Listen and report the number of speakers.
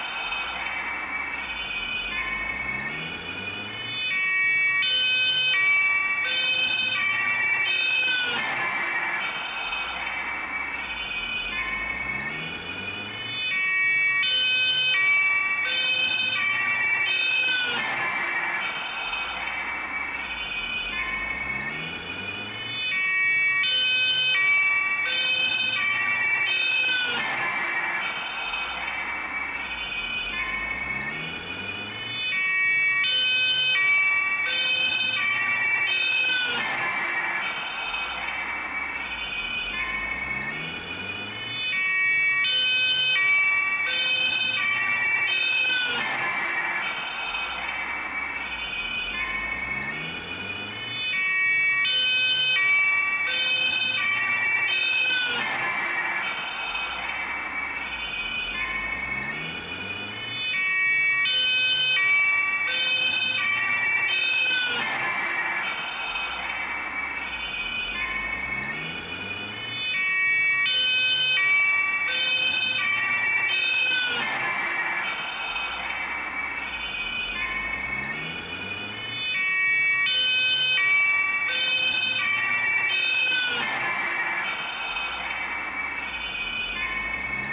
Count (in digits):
0